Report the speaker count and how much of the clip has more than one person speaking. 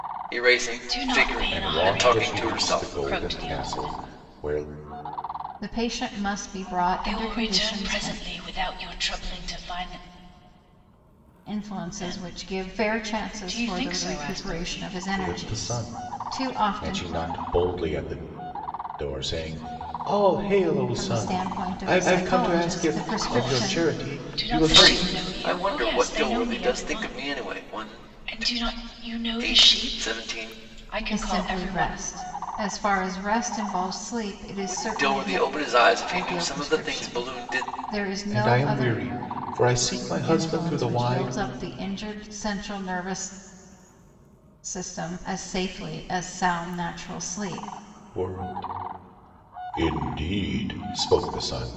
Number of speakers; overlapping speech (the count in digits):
4, about 47%